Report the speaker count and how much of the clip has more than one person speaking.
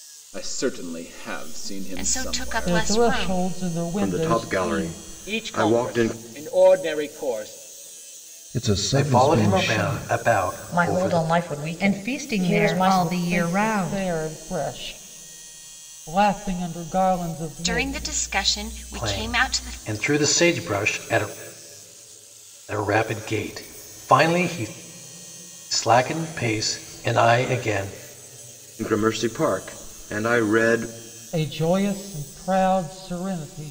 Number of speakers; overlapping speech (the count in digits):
9, about 28%